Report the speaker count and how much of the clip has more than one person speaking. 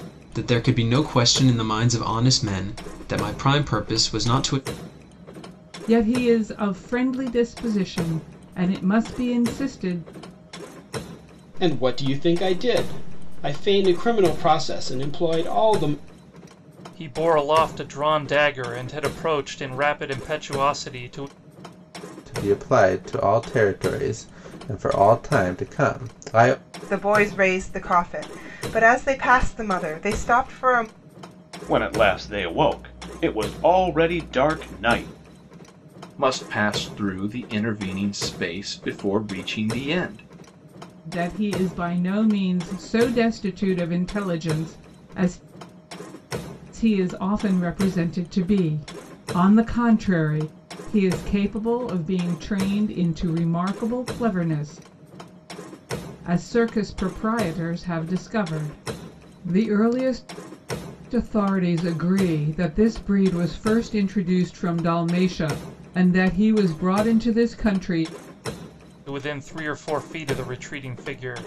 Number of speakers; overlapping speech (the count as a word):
eight, no overlap